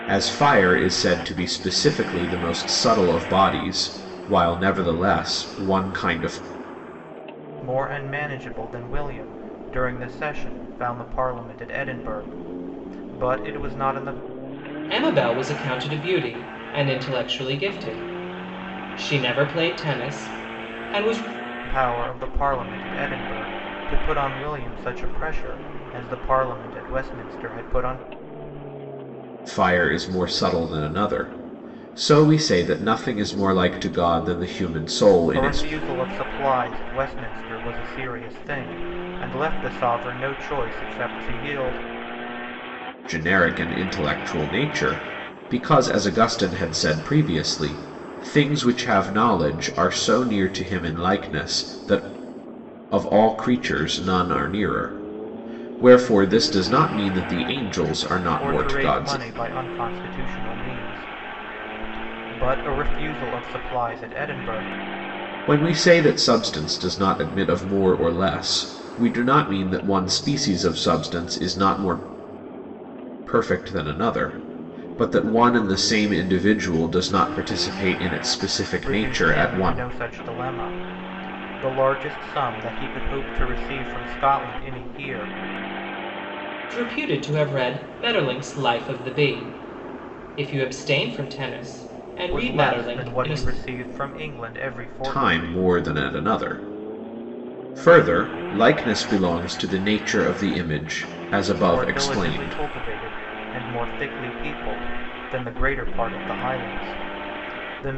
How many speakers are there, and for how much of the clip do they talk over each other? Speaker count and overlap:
3, about 5%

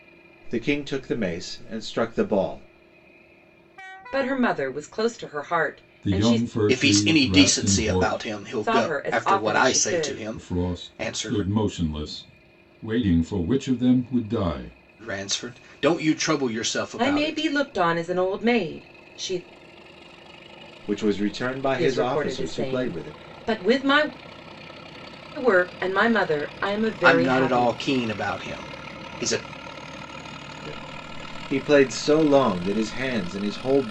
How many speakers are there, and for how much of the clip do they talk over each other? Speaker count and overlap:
4, about 21%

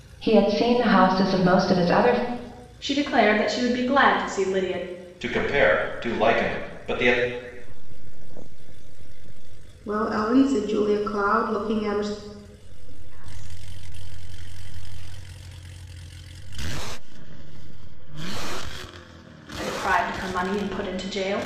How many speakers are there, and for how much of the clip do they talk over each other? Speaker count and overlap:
5, no overlap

